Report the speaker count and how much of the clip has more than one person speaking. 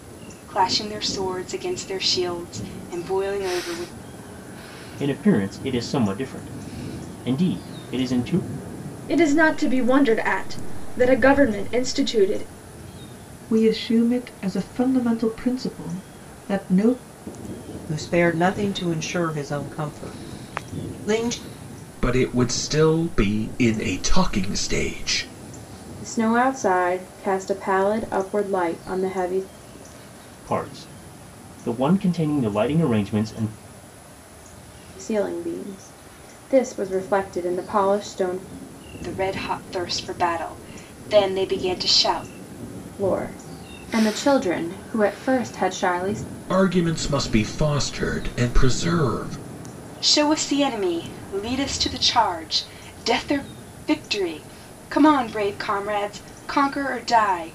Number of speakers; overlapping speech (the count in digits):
7, no overlap